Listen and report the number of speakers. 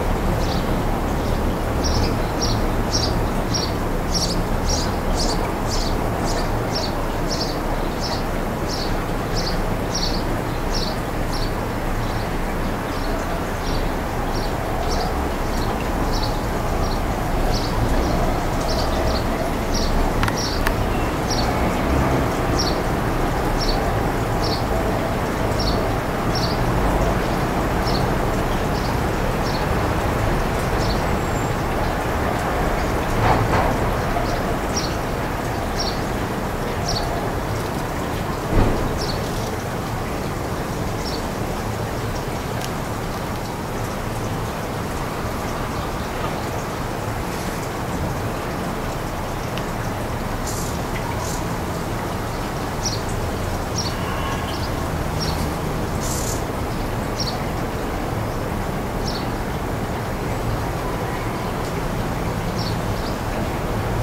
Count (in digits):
0